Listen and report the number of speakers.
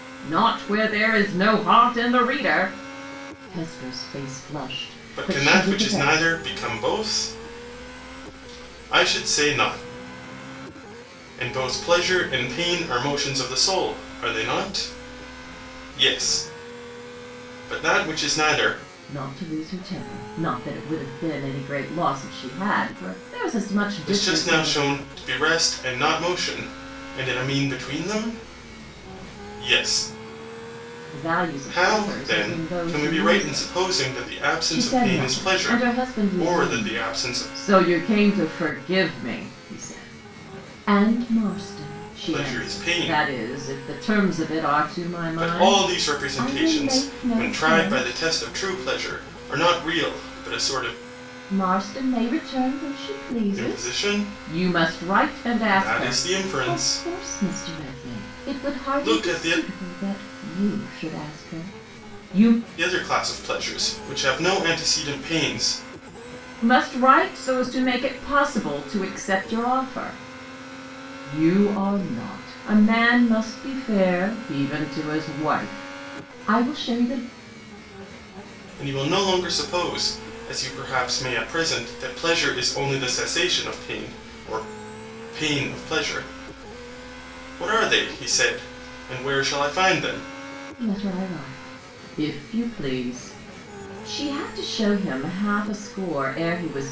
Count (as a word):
two